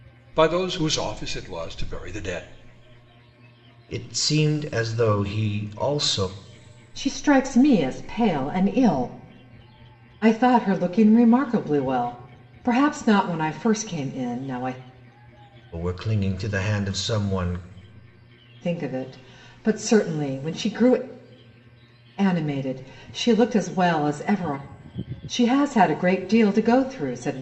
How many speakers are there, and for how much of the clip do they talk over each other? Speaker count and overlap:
three, no overlap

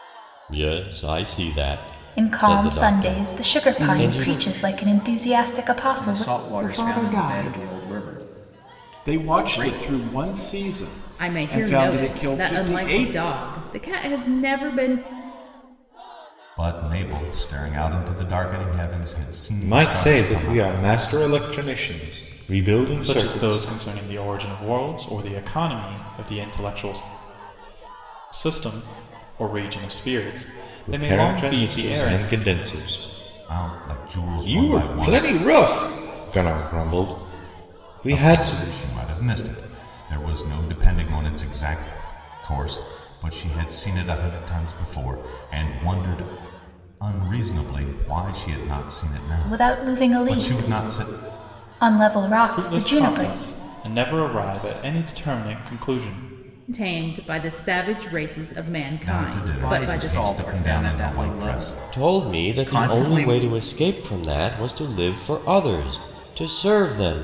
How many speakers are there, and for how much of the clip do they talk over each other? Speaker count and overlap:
nine, about 31%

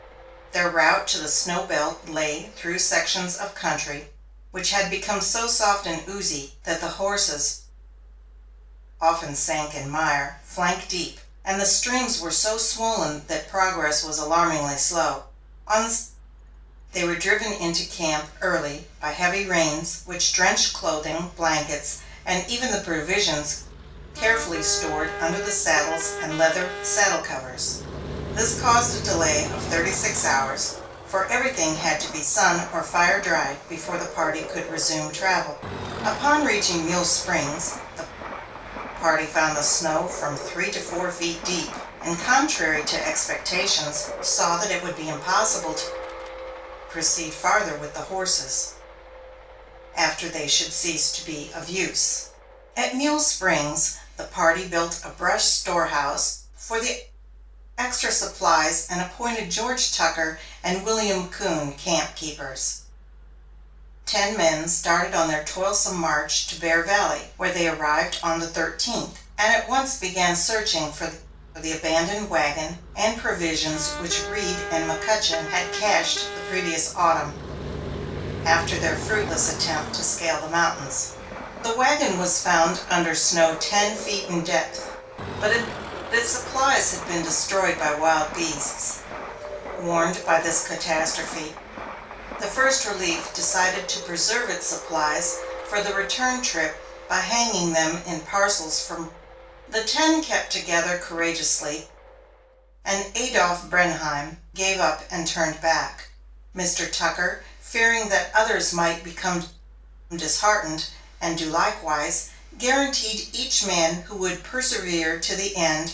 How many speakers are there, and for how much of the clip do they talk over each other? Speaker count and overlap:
one, no overlap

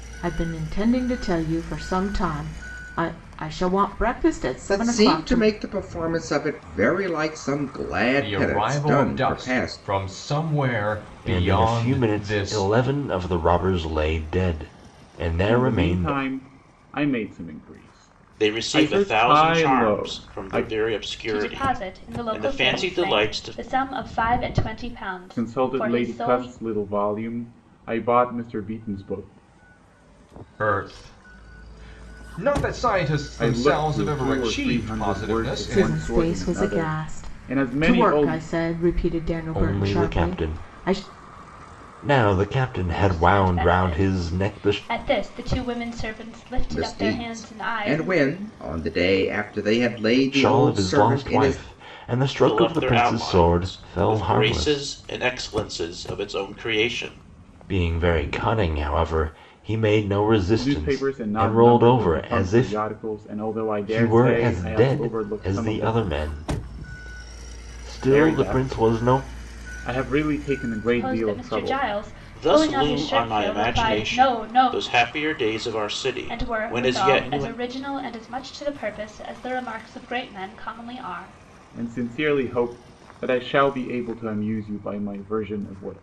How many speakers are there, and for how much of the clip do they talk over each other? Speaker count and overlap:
seven, about 40%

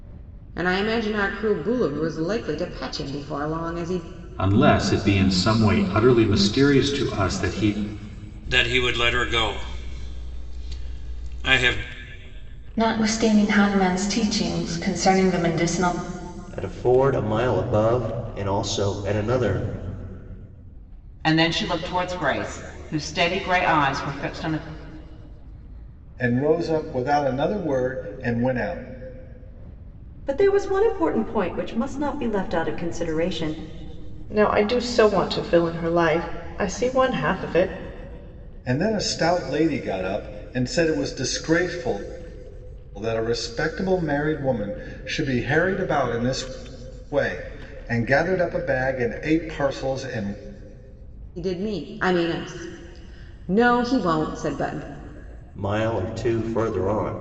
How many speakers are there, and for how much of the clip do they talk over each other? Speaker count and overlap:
nine, no overlap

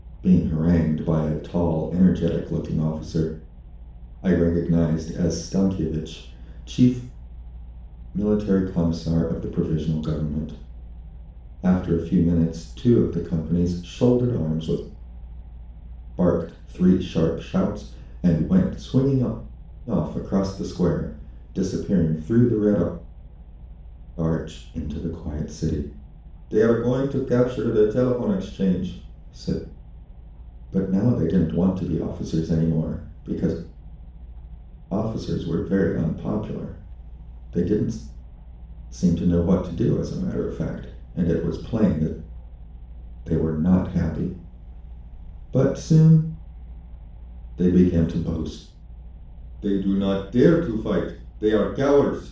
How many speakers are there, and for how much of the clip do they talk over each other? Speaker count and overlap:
one, no overlap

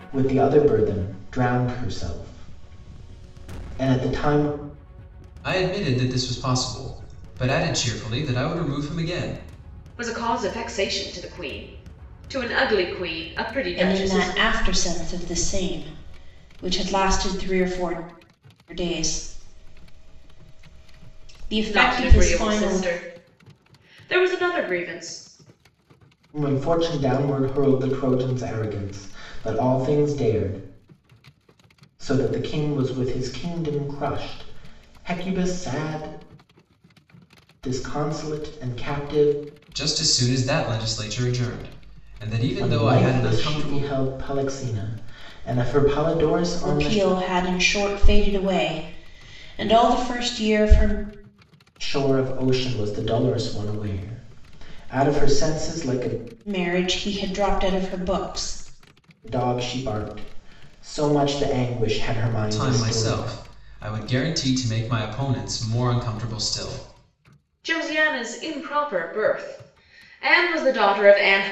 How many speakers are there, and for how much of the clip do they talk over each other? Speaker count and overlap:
four, about 6%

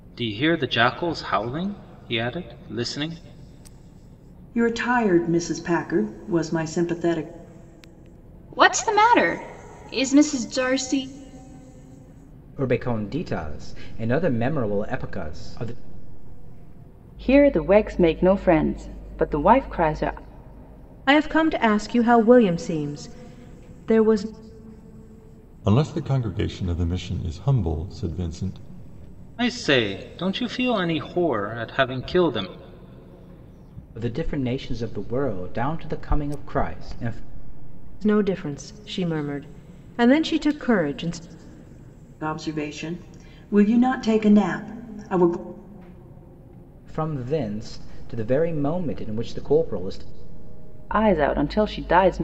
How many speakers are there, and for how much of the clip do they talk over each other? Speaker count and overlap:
seven, no overlap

